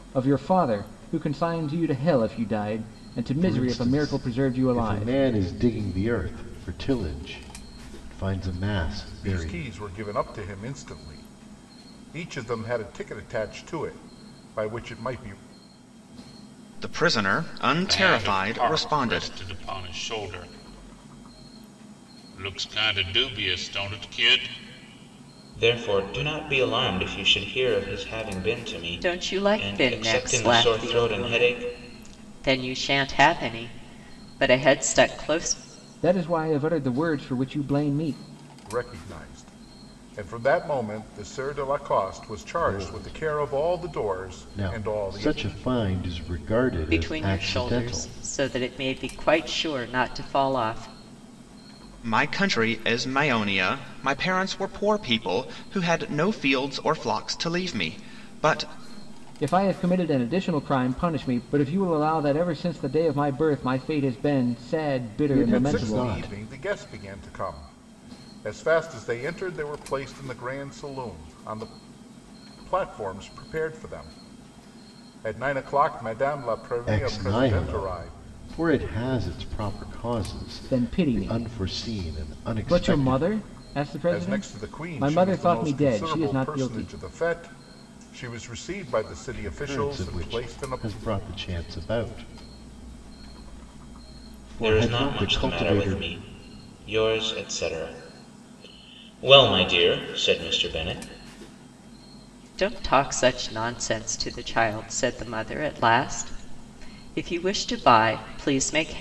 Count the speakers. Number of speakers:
7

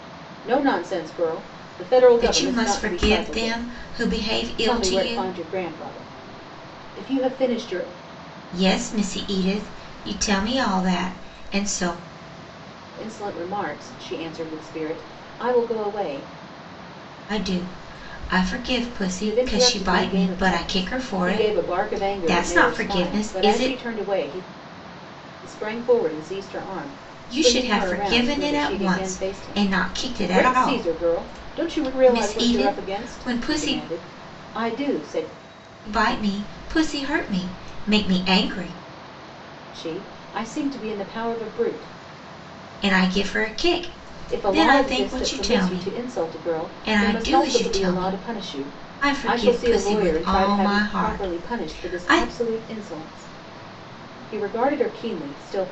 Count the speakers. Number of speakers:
2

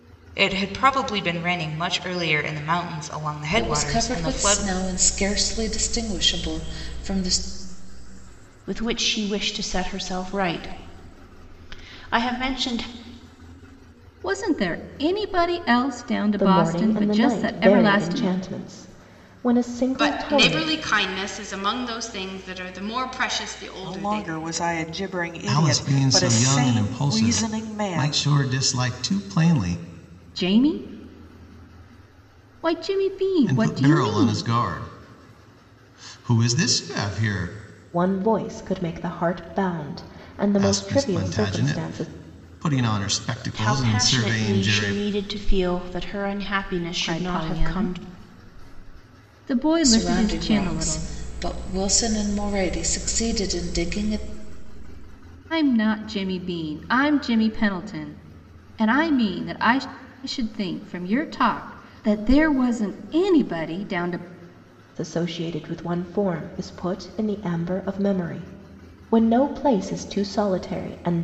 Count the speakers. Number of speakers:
8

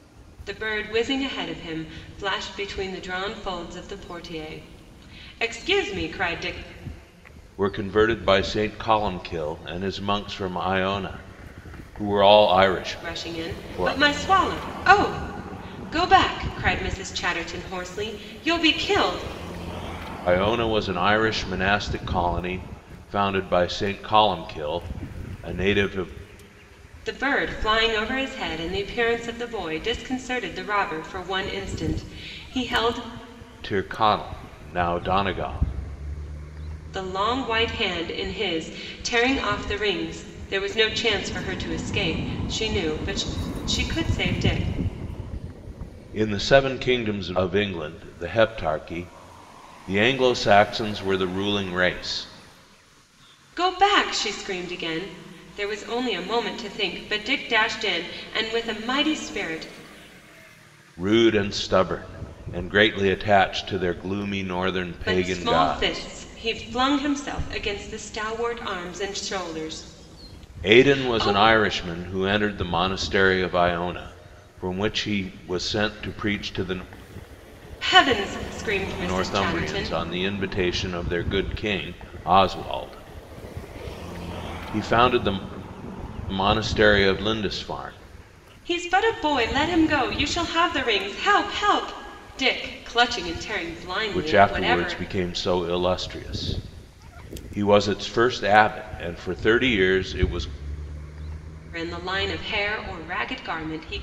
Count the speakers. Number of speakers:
2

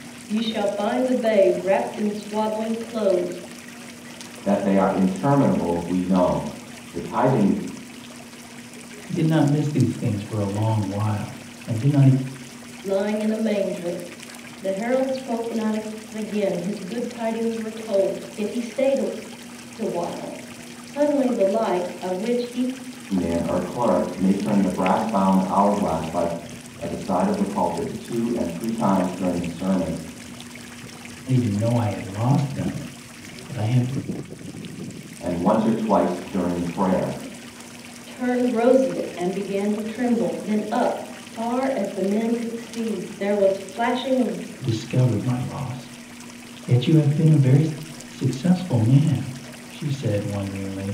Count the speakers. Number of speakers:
3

